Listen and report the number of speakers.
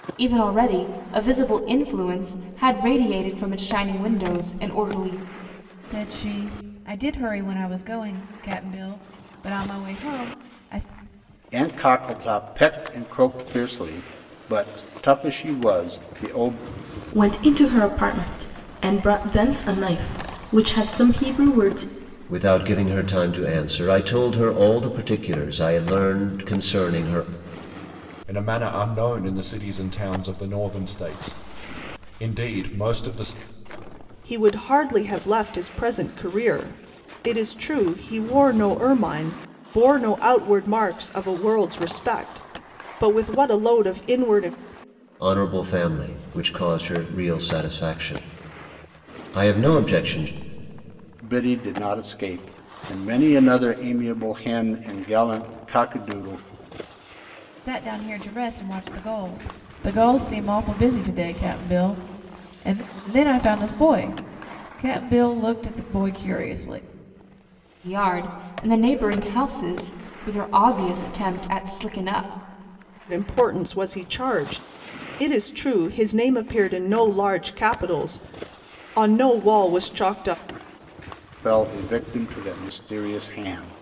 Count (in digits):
7